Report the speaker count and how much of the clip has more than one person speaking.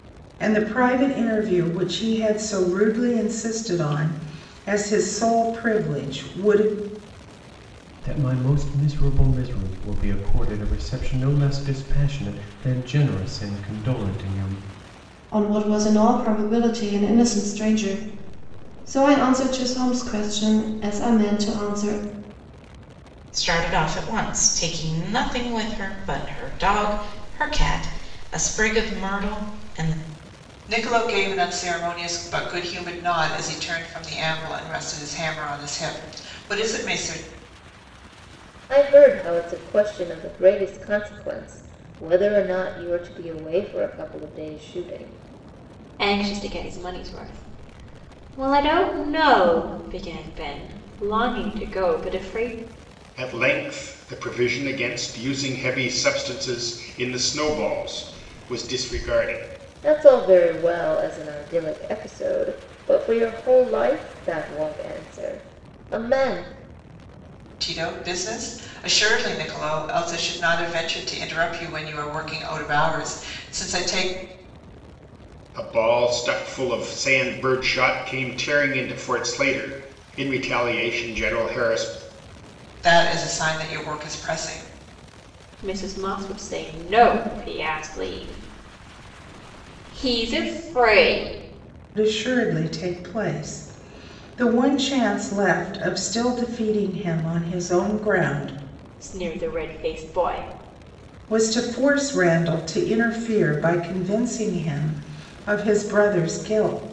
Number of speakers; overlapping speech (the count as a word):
eight, no overlap